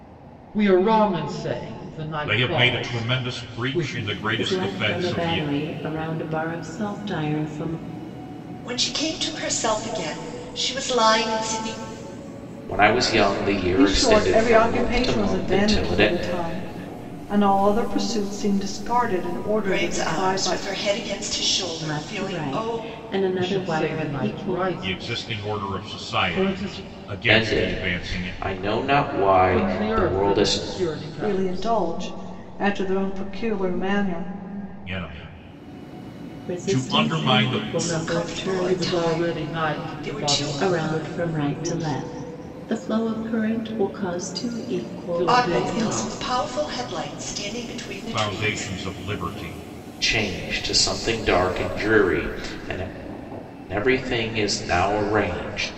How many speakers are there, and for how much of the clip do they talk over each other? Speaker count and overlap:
6, about 37%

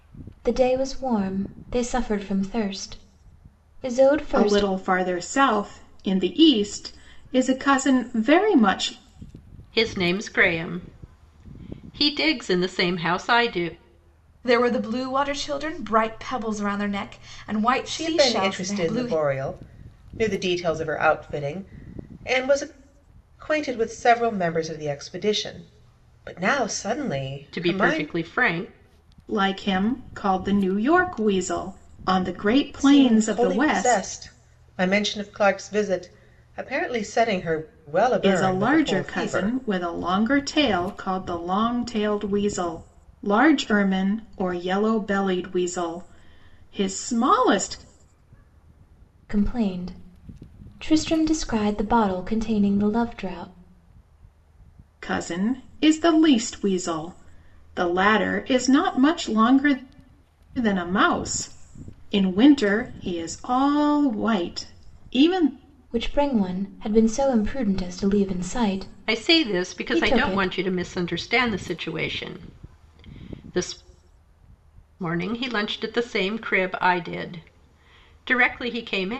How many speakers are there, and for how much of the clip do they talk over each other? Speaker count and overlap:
5, about 8%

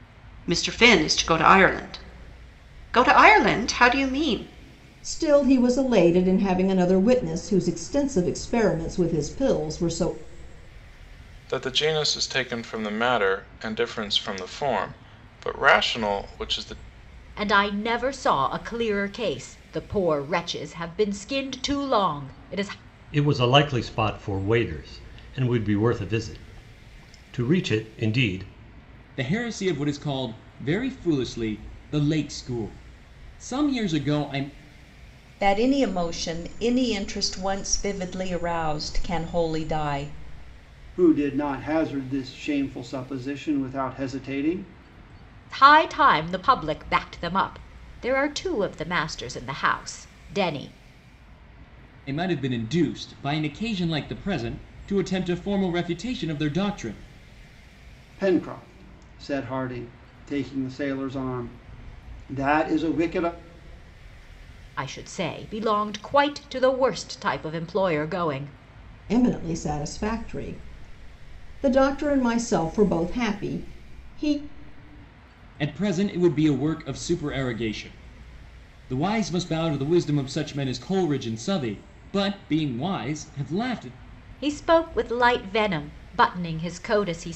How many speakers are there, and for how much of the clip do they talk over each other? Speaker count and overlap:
8, no overlap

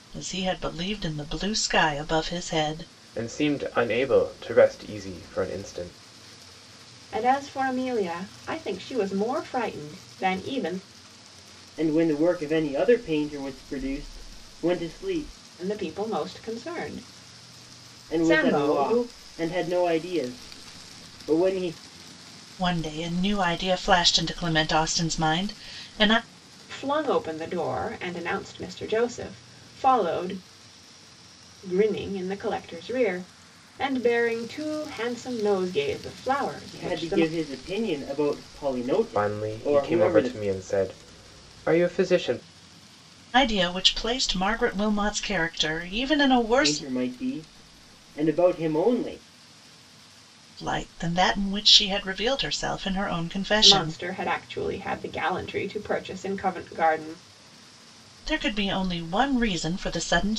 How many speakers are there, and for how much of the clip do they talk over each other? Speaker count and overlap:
4, about 6%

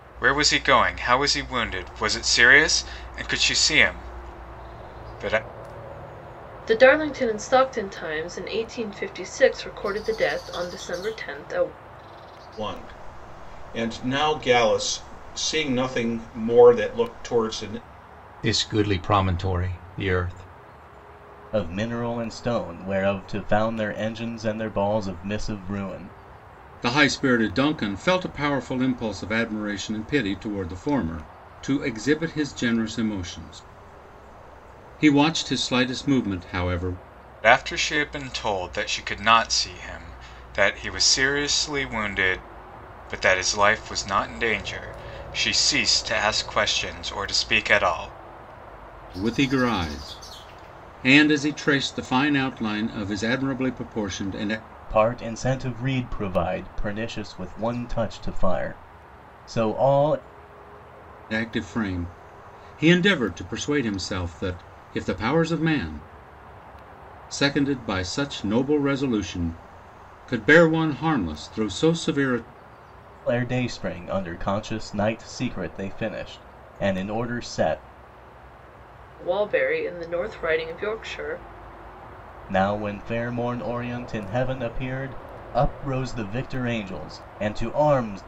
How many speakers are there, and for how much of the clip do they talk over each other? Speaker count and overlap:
6, no overlap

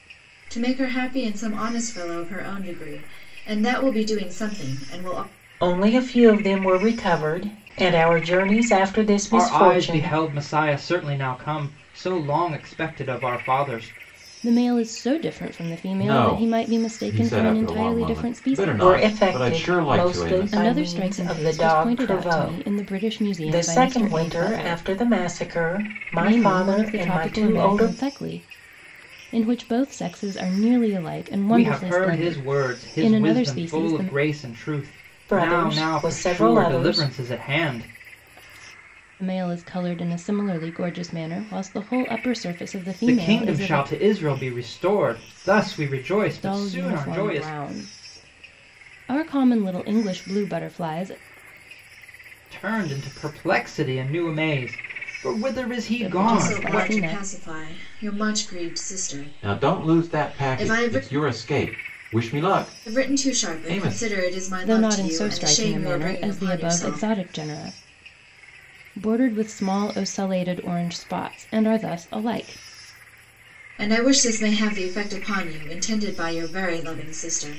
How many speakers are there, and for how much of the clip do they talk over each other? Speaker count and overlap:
5, about 31%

